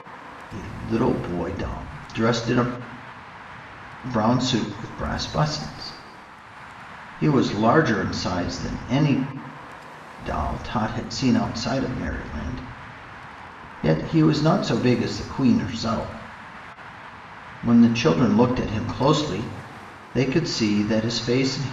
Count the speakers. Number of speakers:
one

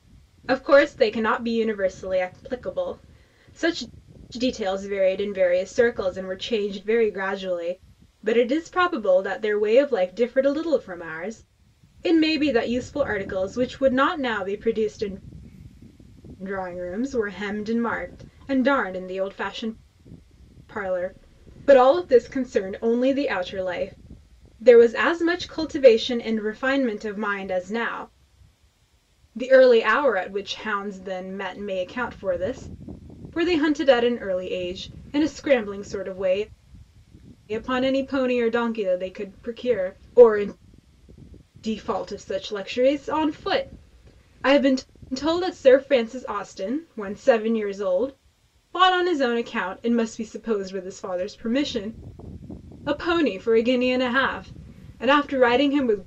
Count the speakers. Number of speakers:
one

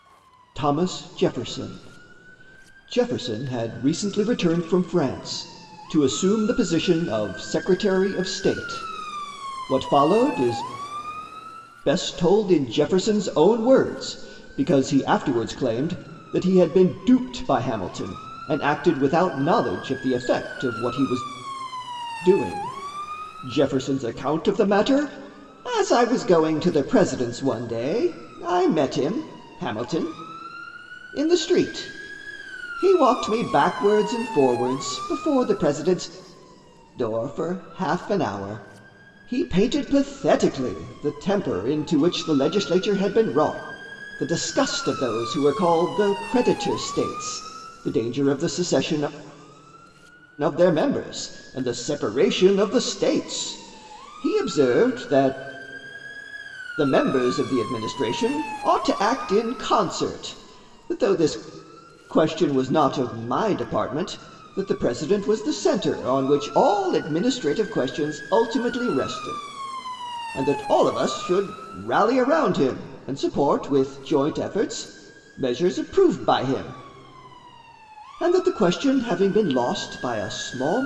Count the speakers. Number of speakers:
one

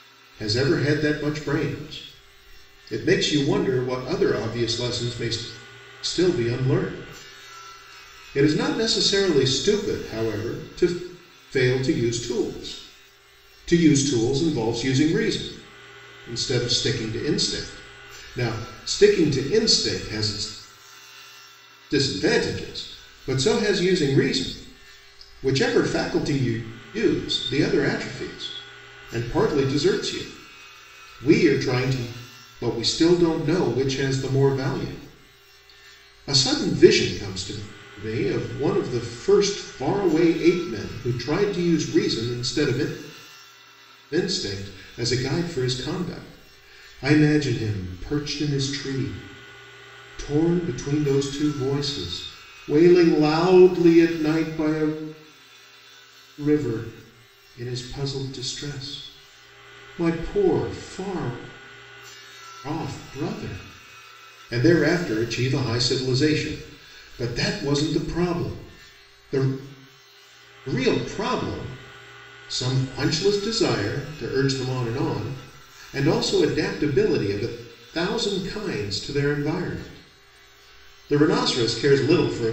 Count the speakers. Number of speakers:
one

